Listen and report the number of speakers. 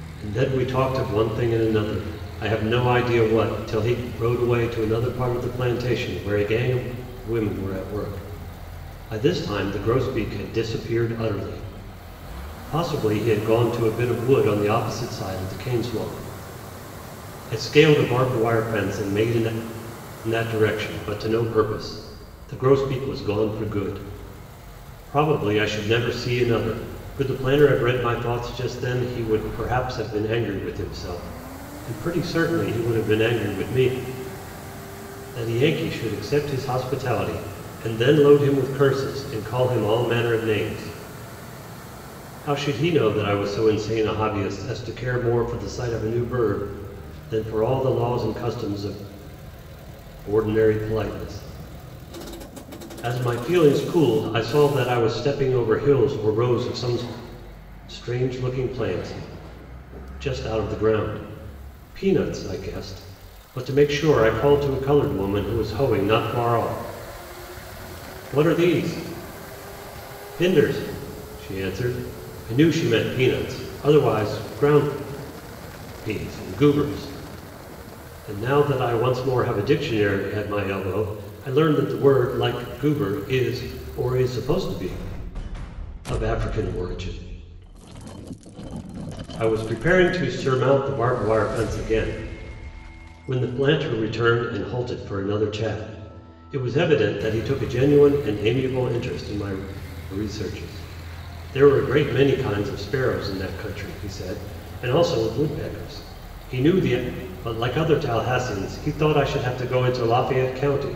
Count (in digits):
1